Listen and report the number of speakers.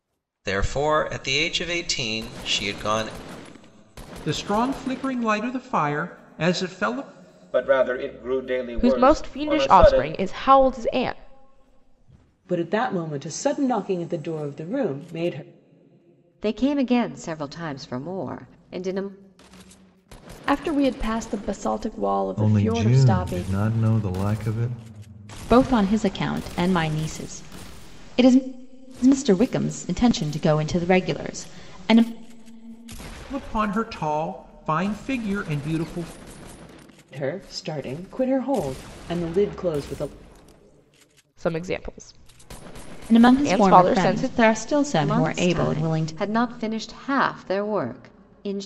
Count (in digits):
9